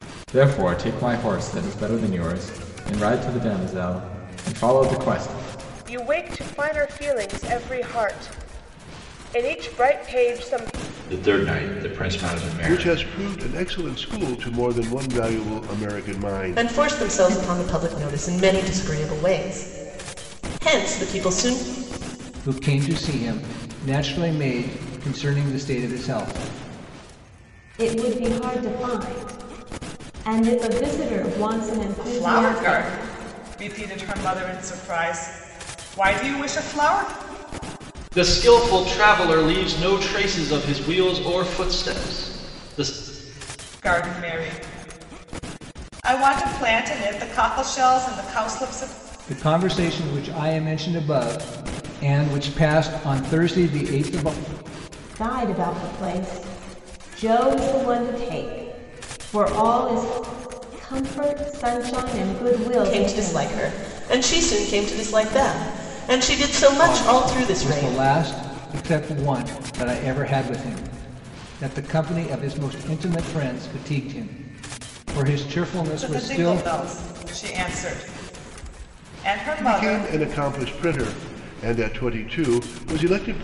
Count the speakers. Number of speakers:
9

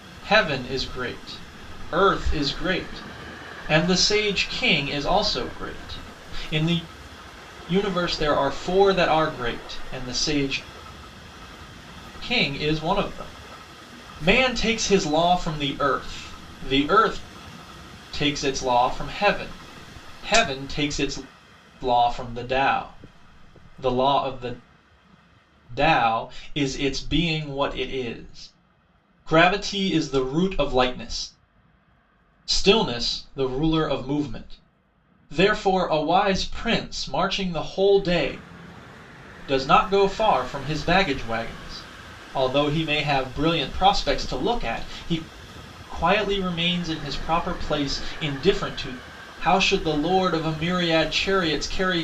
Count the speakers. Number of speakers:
1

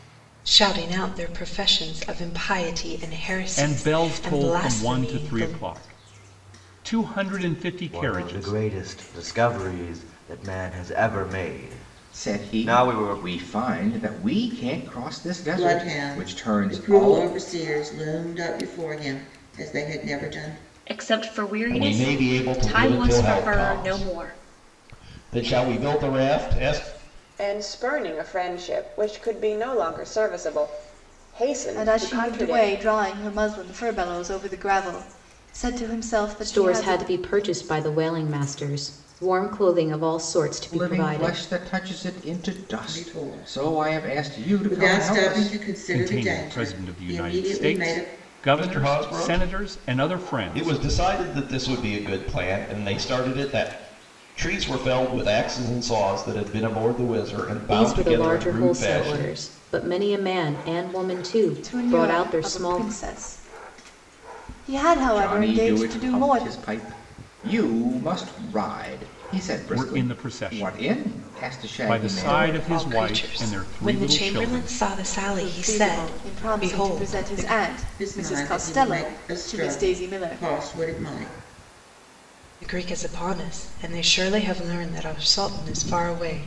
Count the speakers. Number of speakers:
10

